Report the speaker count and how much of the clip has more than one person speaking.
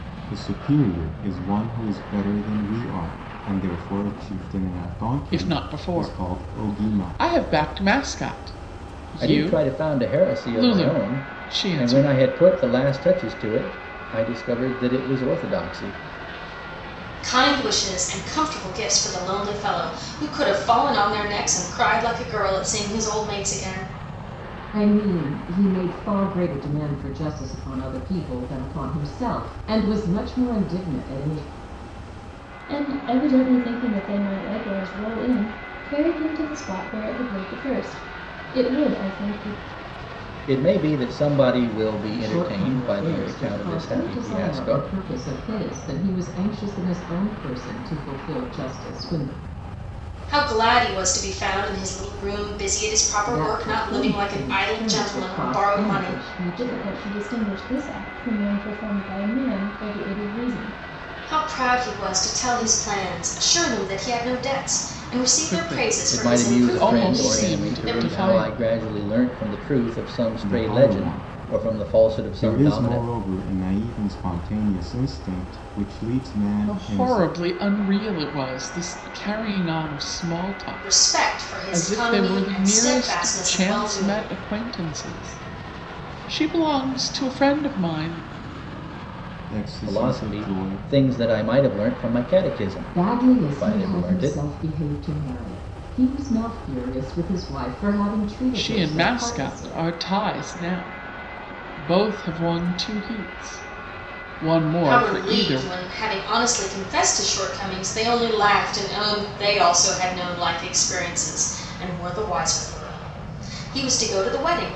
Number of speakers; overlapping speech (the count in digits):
6, about 23%